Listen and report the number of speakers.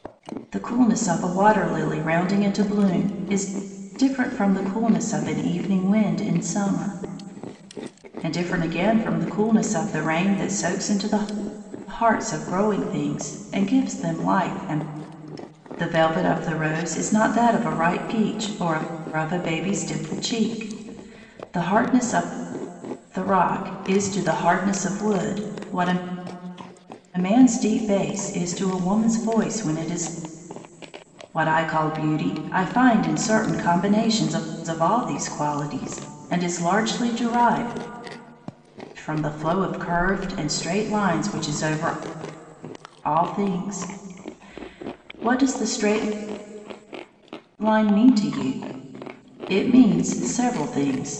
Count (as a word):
one